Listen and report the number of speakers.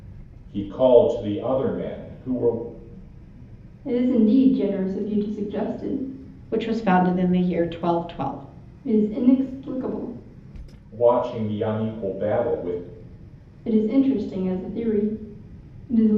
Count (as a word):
three